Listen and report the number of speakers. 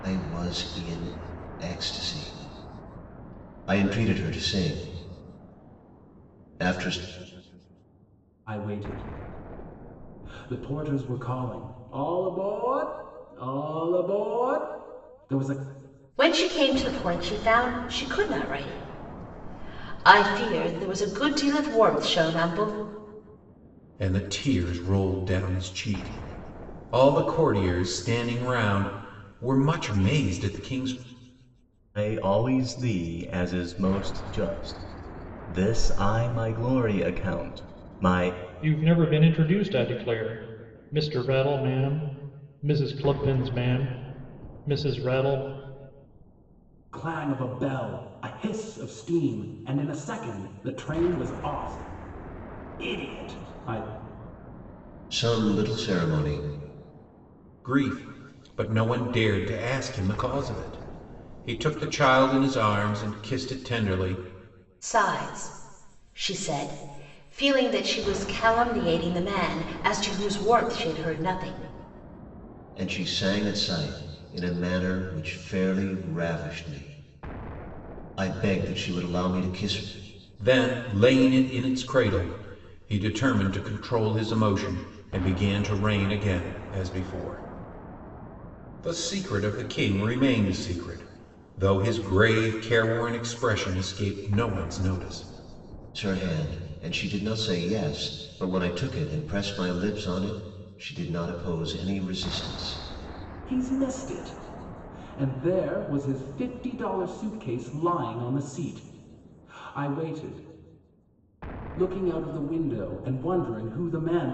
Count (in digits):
6